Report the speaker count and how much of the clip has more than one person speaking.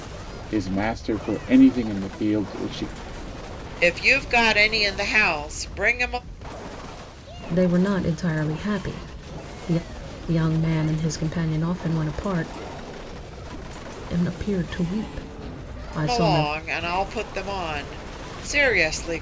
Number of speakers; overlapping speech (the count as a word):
three, about 2%